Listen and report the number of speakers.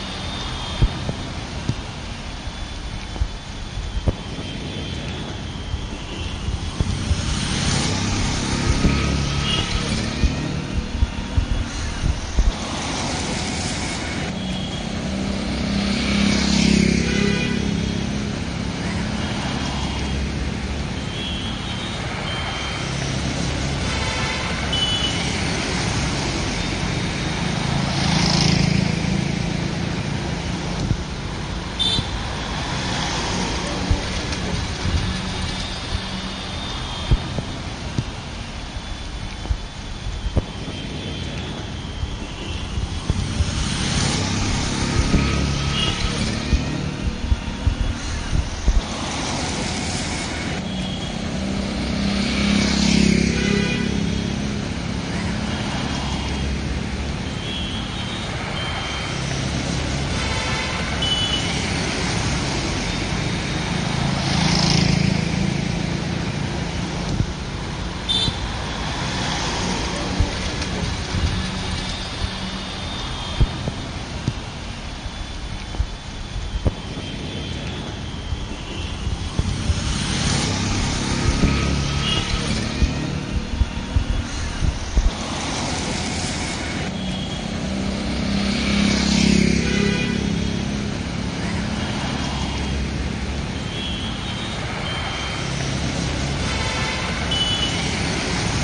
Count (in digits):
0